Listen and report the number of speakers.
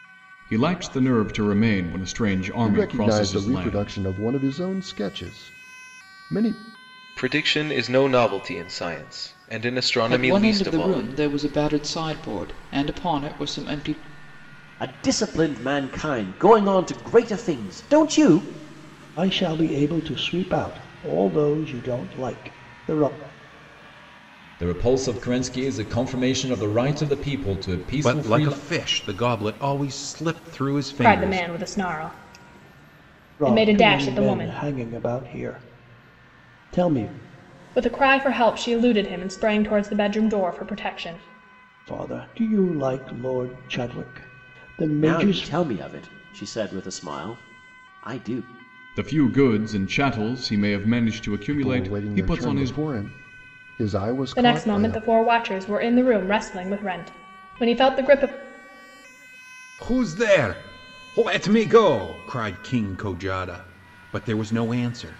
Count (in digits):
9